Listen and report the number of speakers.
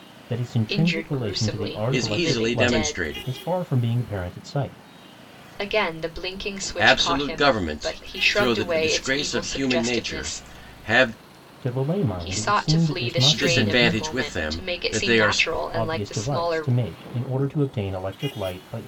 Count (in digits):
3